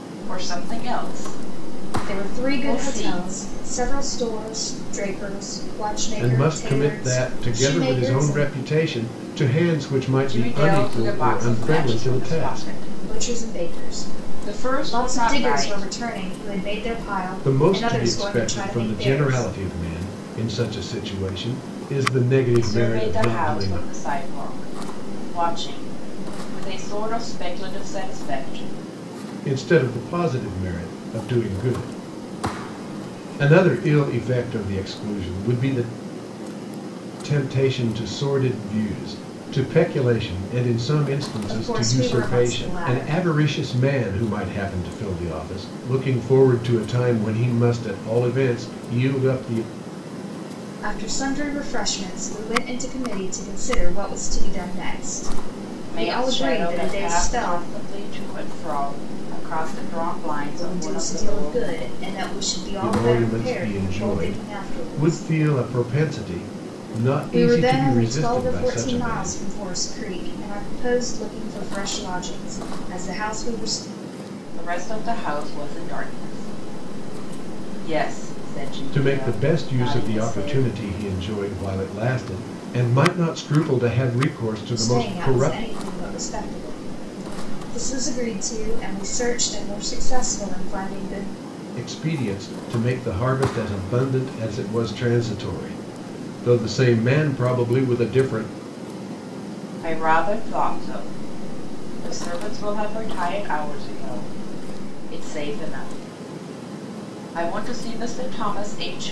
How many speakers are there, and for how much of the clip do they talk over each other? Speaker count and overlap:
3, about 23%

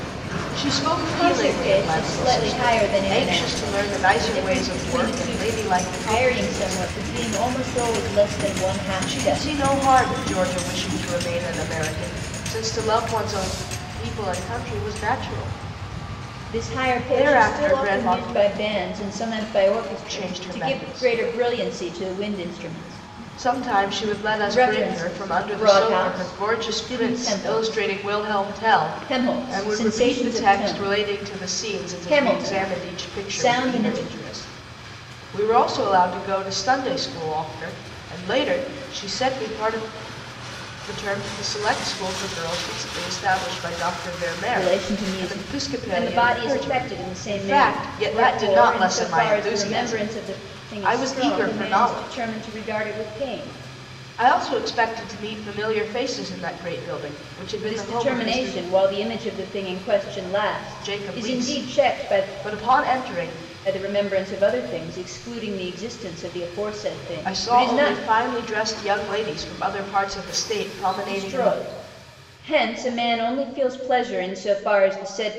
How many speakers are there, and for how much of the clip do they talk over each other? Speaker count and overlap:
2, about 40%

